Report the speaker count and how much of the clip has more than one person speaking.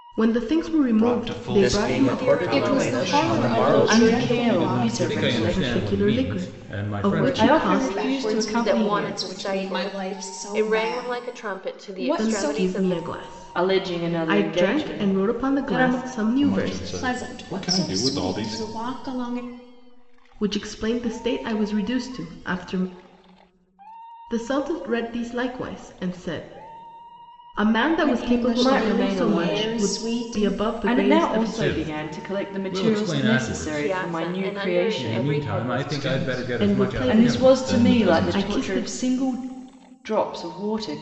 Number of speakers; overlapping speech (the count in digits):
8, about 68%